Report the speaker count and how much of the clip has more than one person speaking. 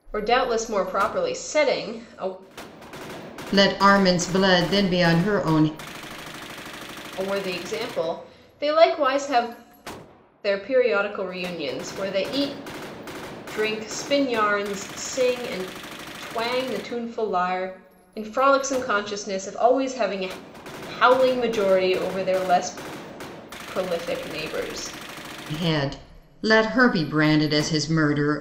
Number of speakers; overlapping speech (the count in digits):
2, no overlap